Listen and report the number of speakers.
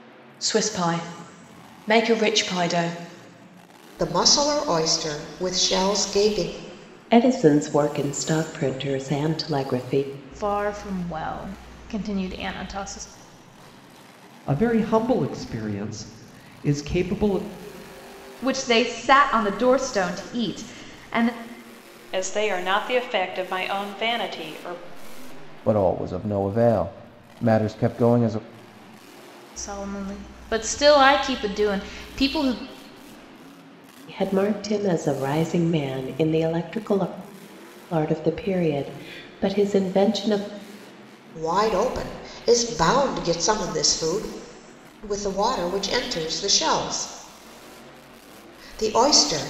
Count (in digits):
8